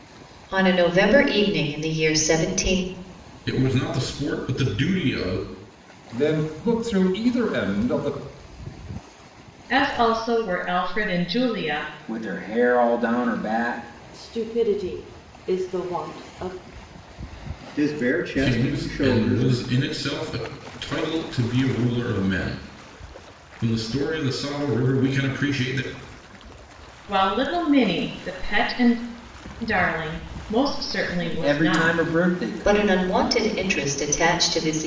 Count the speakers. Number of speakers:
seven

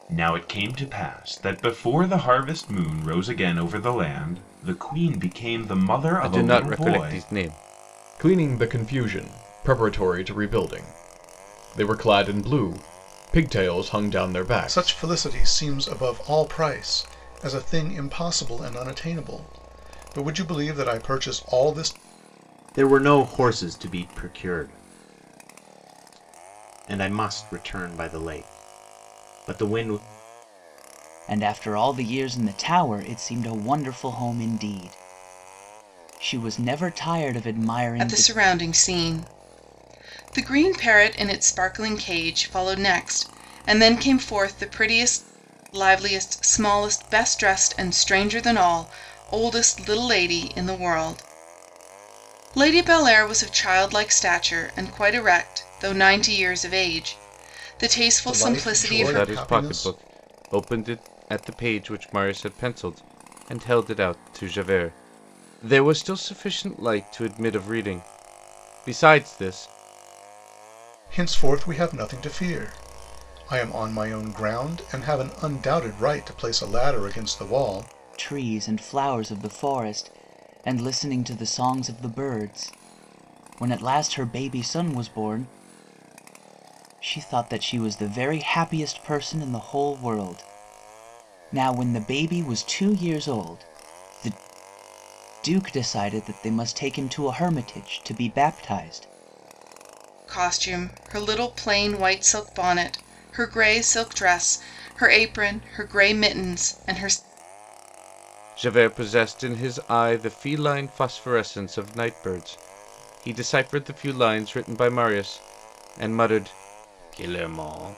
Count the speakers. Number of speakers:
seven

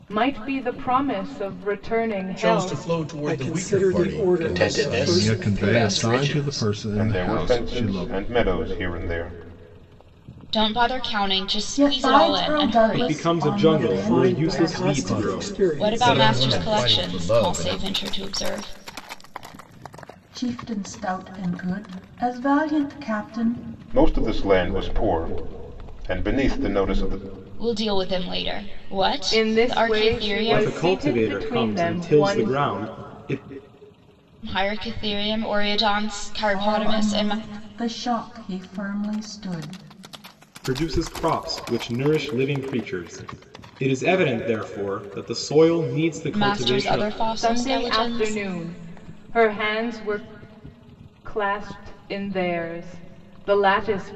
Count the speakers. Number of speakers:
nine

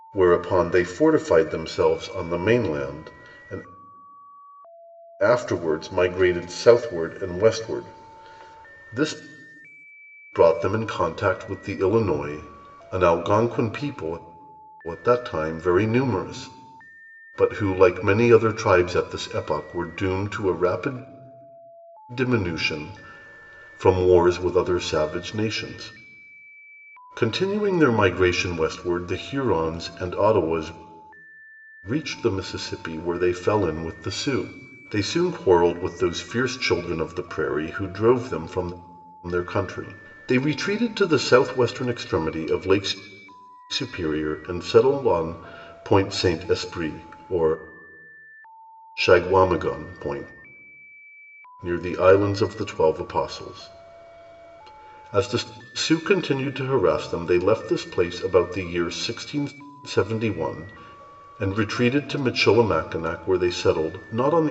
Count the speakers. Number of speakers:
one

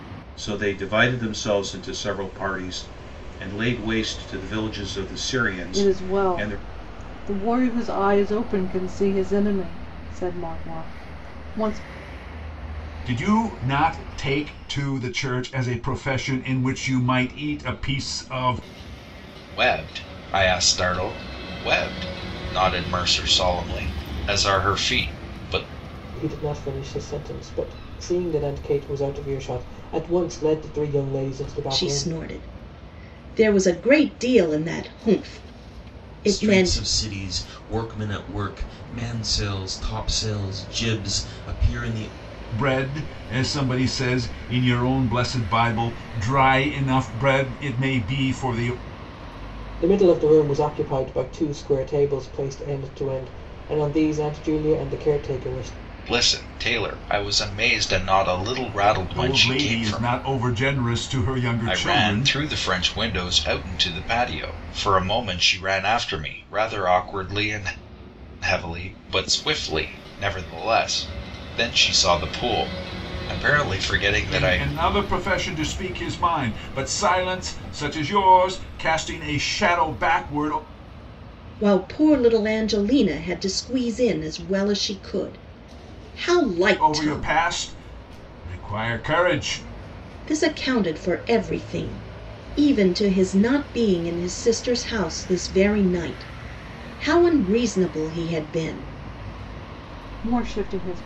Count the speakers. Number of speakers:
seven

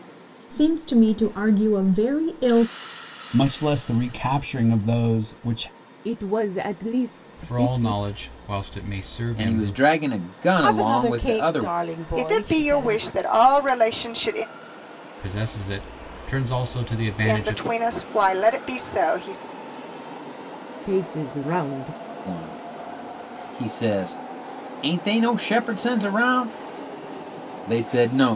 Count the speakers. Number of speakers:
seven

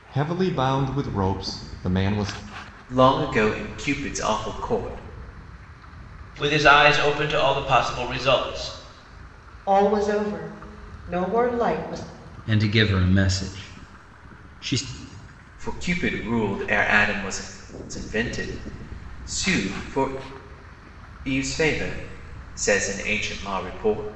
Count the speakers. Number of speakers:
five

